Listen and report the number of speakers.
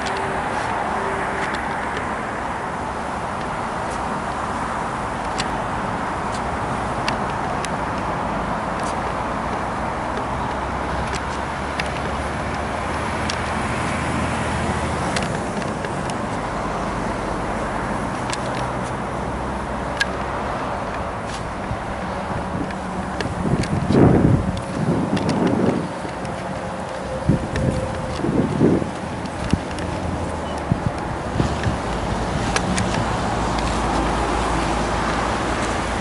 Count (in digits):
0